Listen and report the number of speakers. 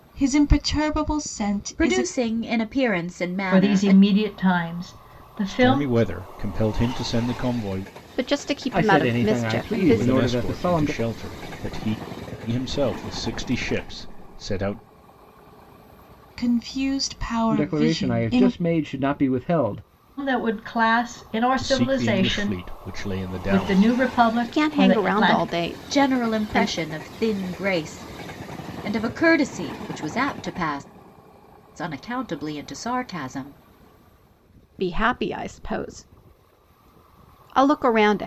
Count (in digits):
6